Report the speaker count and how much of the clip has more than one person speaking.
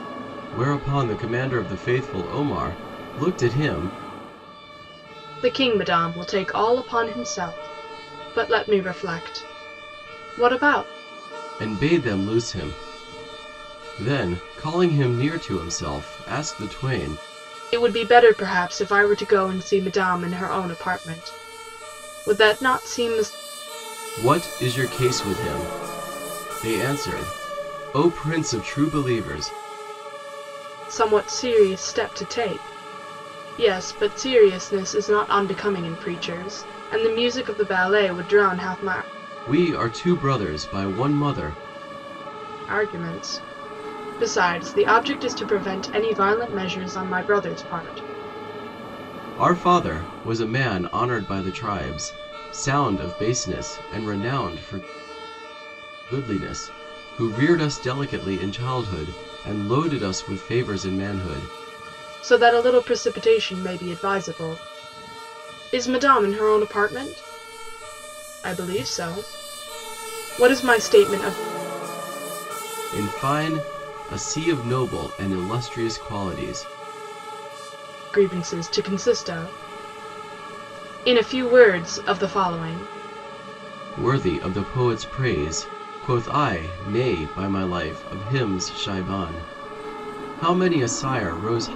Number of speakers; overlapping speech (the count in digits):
2, no overlap